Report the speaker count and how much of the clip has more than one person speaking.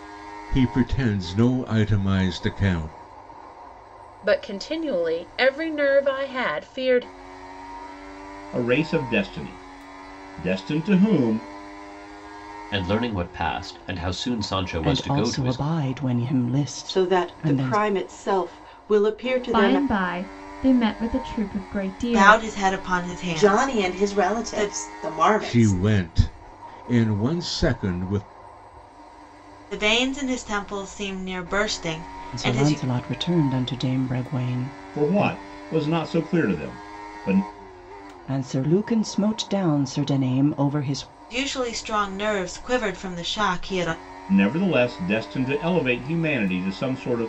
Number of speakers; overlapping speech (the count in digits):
9, about 11%